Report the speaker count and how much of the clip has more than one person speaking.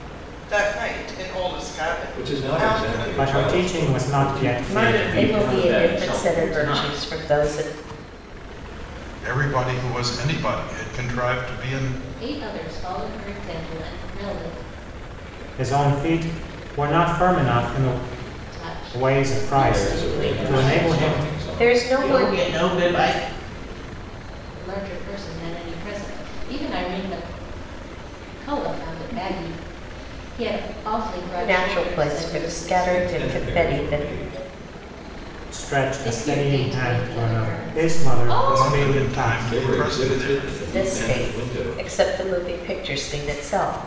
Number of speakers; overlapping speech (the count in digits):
7, about 39%